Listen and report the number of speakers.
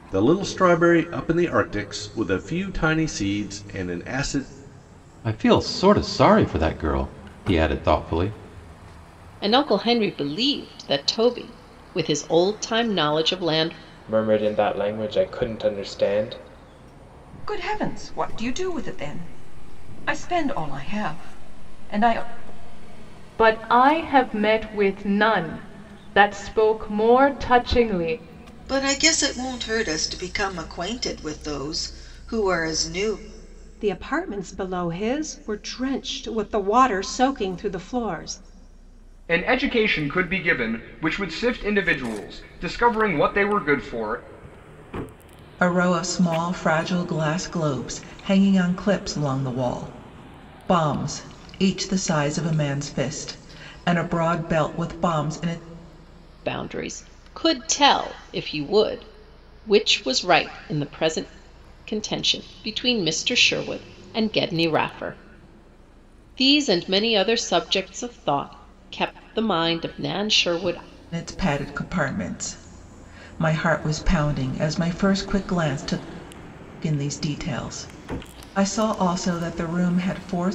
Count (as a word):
ten